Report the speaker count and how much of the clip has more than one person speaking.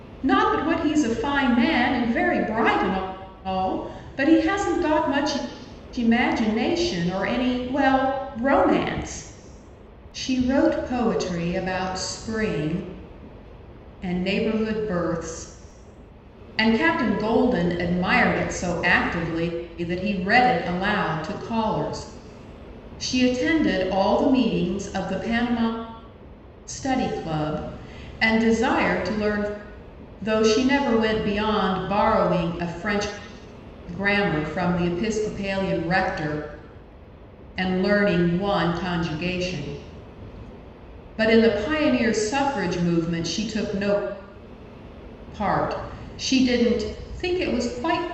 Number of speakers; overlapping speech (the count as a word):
one, no overlap